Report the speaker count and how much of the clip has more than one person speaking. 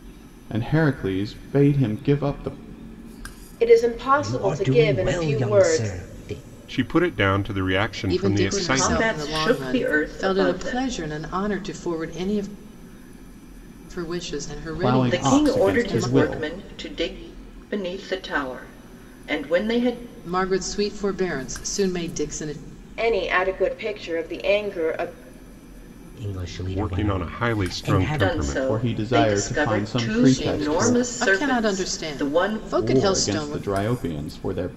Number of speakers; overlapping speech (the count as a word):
six, about 37%